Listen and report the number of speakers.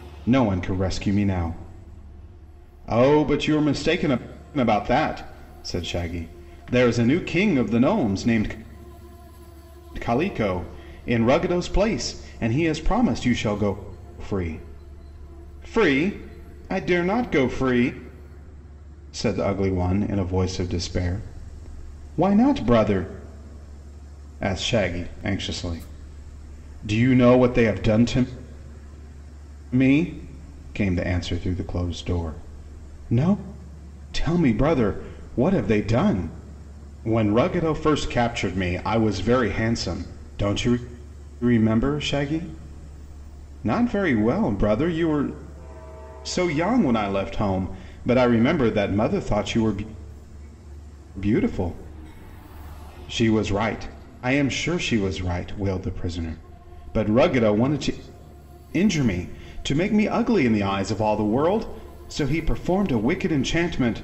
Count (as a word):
one